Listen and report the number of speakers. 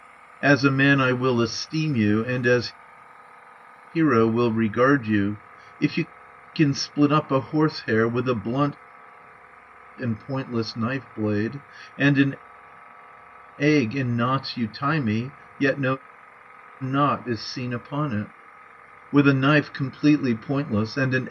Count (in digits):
1